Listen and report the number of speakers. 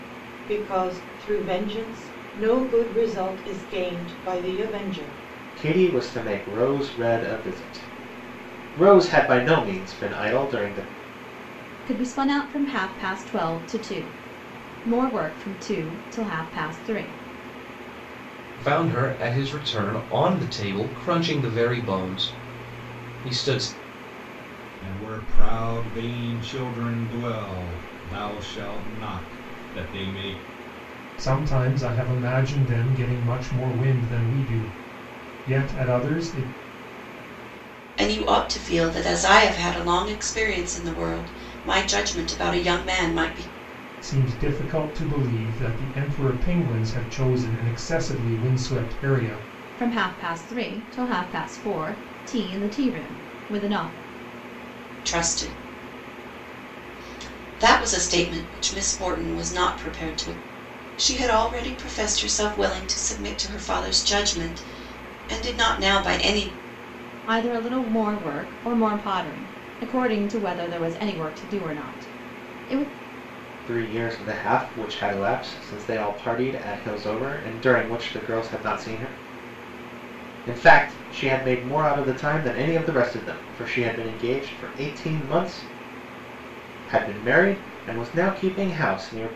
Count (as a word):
seven